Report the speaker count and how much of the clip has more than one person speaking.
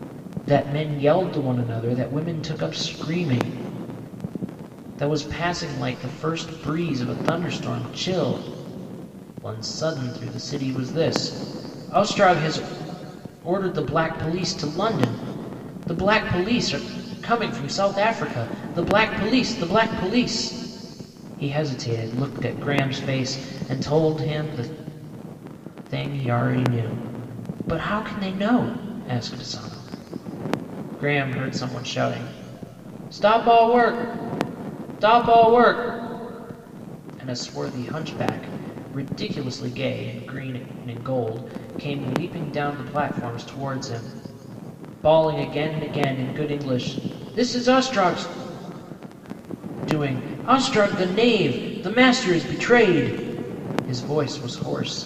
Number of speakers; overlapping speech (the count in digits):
1, no overlap